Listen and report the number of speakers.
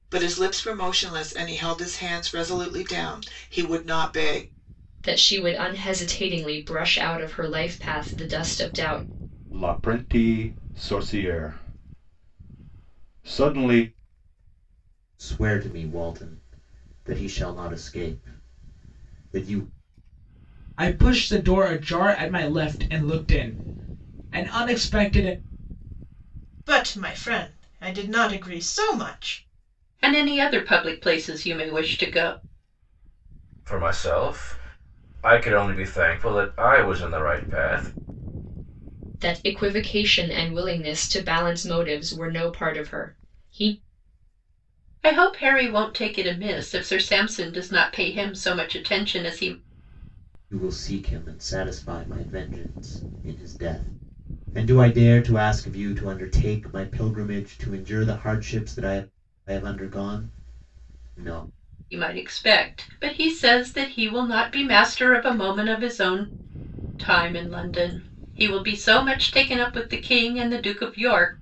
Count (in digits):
8